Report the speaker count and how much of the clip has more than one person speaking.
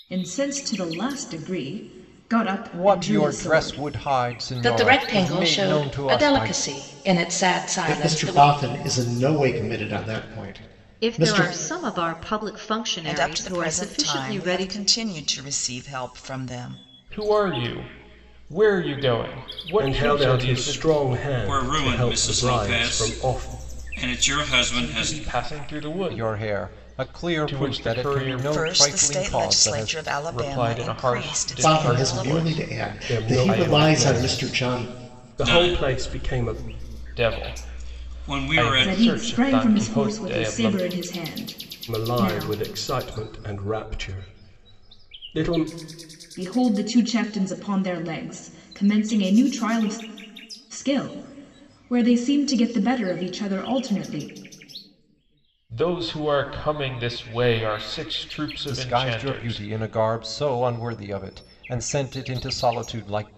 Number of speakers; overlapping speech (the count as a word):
nine, about 39%